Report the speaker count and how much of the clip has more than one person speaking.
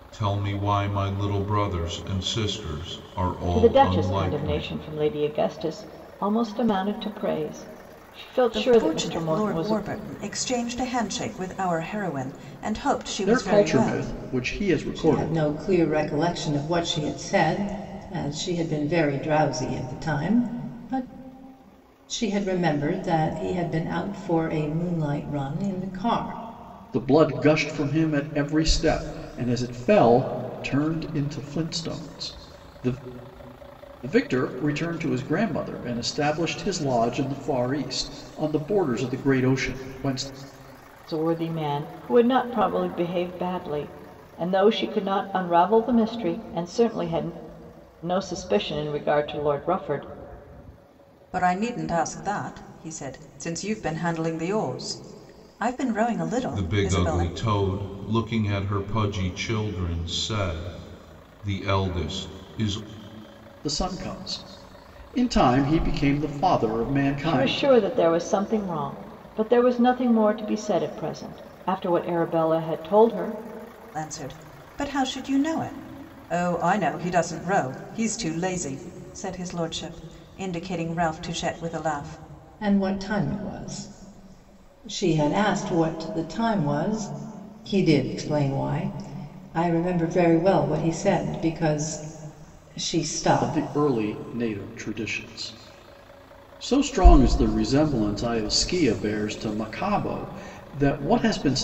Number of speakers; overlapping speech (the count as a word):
five, about 6%